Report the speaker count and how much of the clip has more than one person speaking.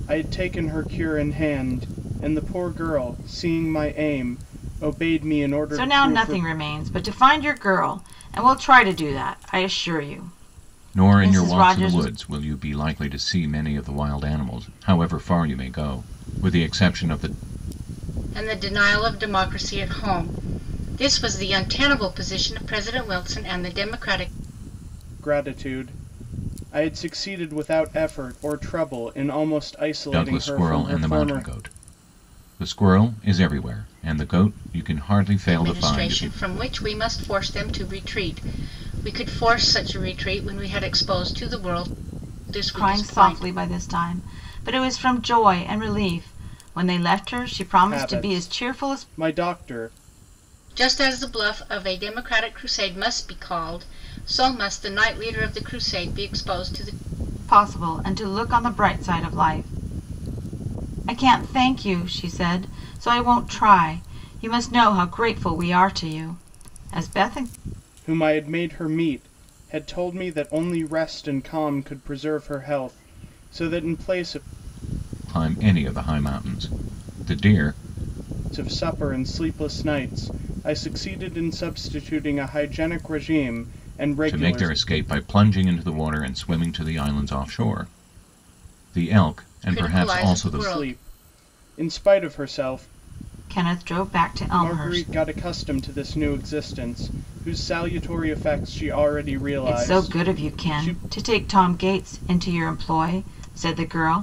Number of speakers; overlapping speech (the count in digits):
4, about 10%